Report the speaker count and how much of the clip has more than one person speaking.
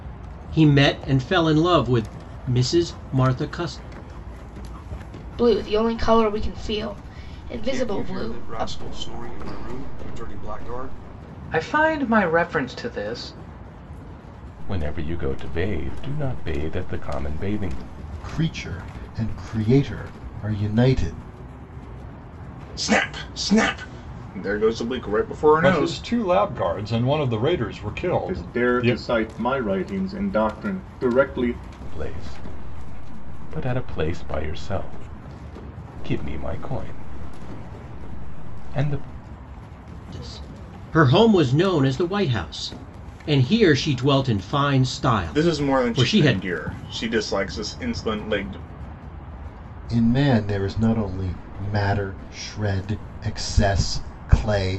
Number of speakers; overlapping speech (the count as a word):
nine, about 7%